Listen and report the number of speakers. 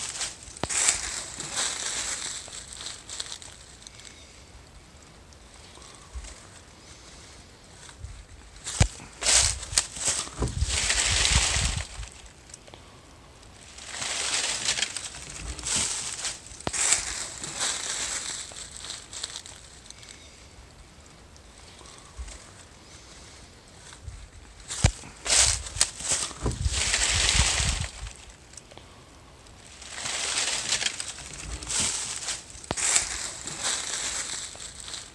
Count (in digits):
0